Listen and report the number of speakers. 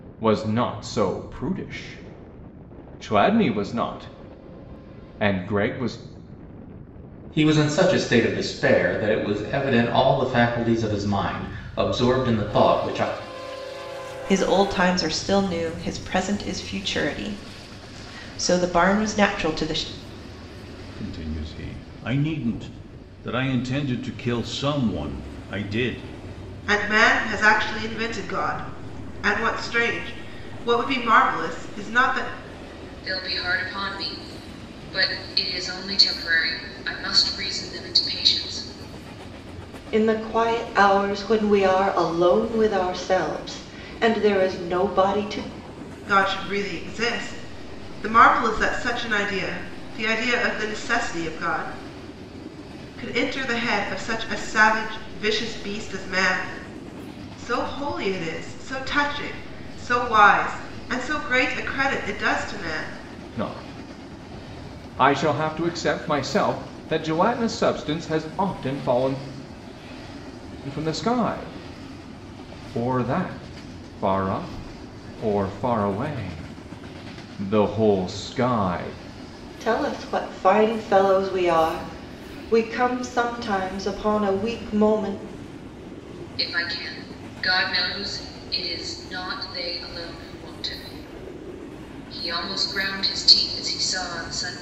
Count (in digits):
7